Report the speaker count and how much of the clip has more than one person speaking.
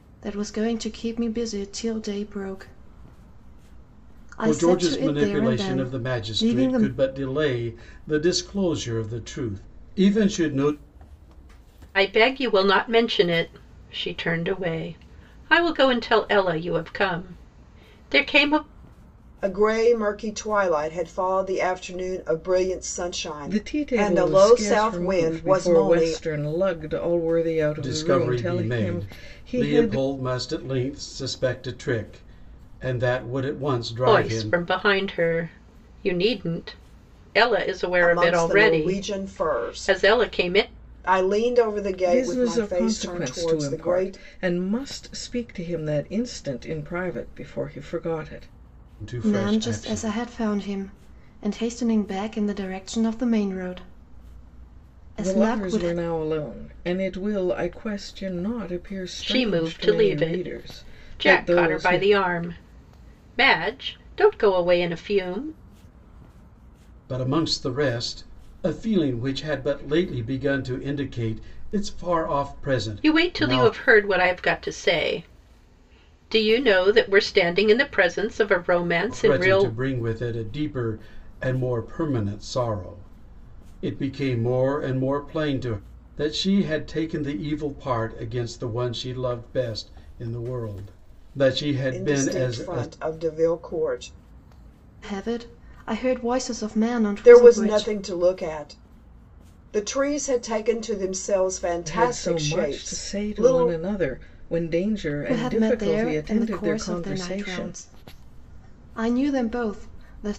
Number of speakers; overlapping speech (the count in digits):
5, about 23%